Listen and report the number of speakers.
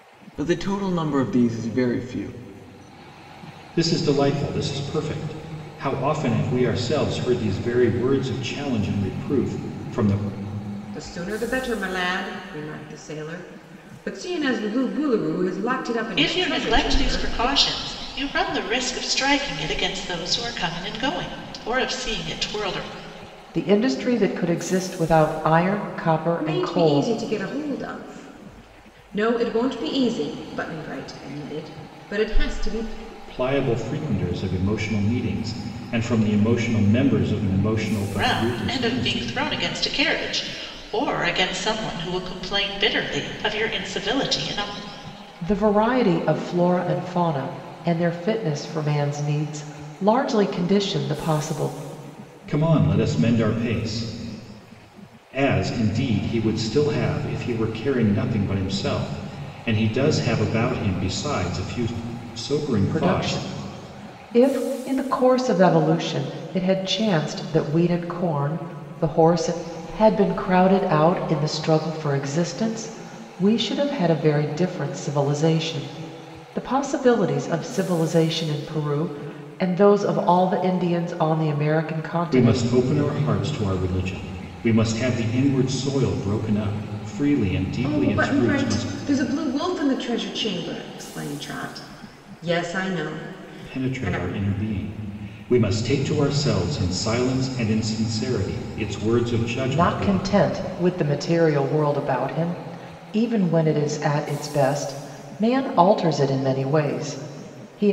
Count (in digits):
5